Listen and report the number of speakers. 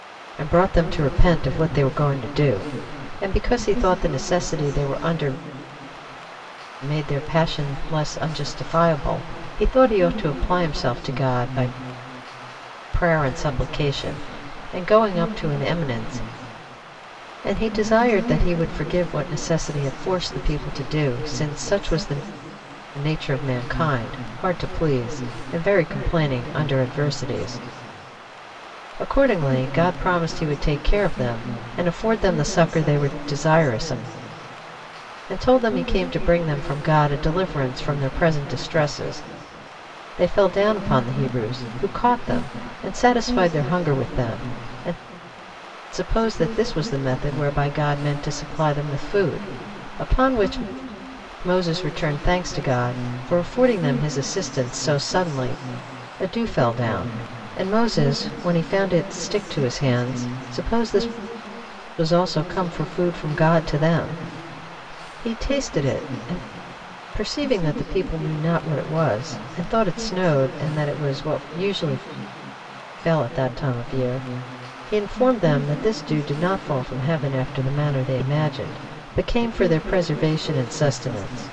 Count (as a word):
one